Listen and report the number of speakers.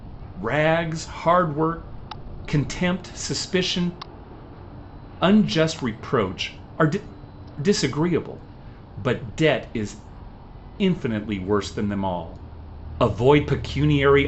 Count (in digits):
1